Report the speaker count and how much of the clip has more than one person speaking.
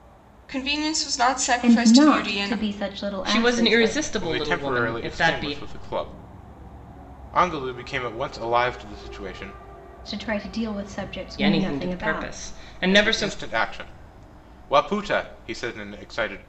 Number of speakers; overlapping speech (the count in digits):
4, about 29%